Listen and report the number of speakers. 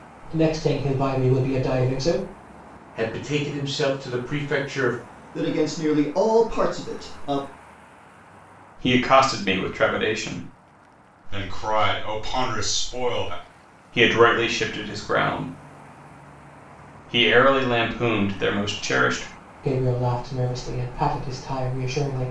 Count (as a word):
five